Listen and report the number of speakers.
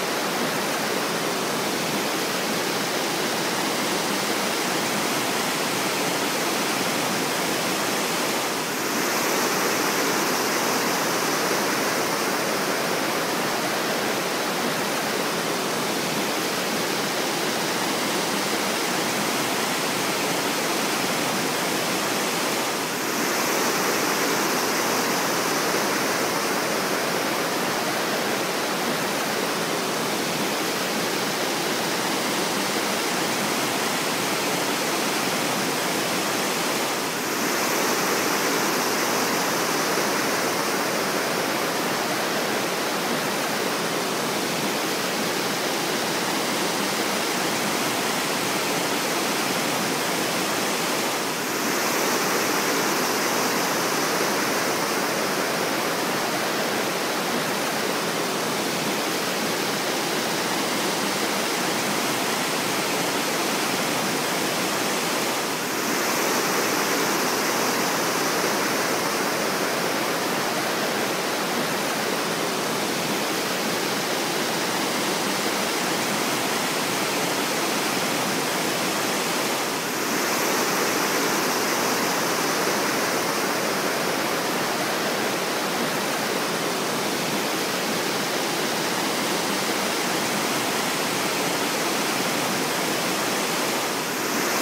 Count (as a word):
zero